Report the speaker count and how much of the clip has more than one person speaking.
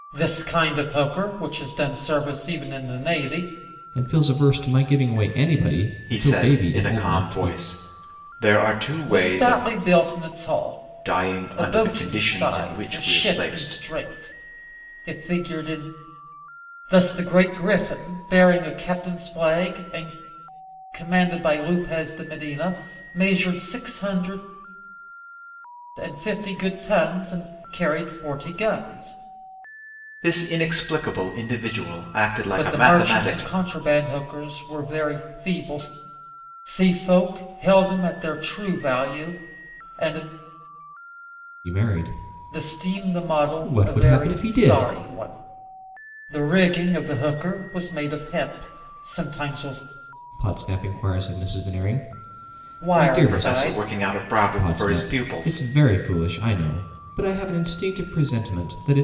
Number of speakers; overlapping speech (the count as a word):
three, about 18%